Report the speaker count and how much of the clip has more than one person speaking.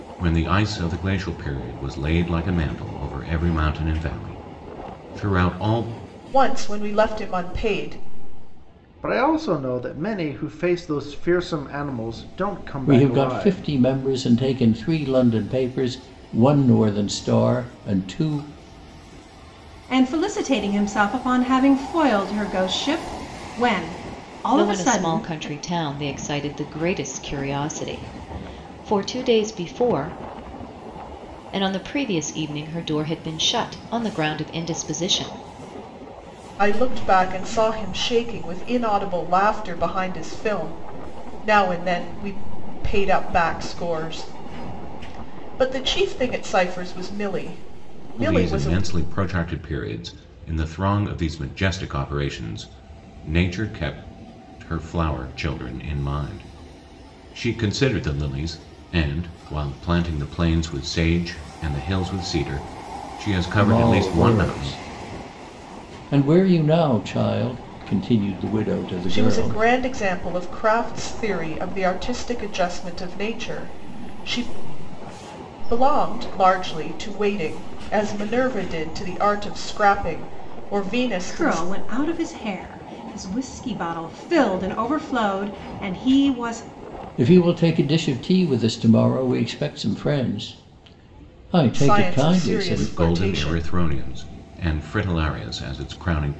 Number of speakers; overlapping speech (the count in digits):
6, about 7%